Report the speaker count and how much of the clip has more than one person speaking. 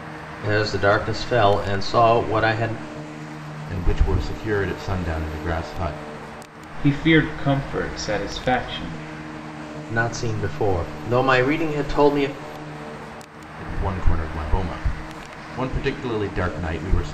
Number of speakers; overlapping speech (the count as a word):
three, no overlap